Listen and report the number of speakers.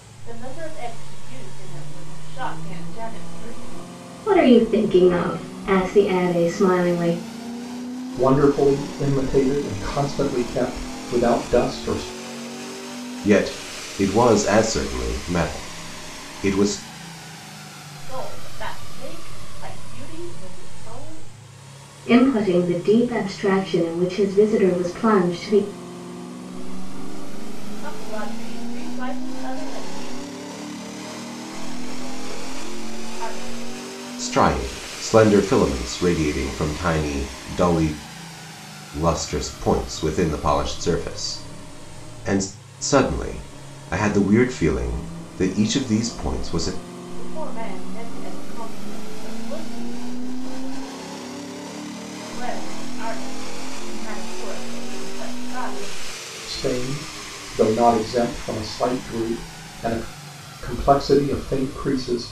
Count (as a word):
four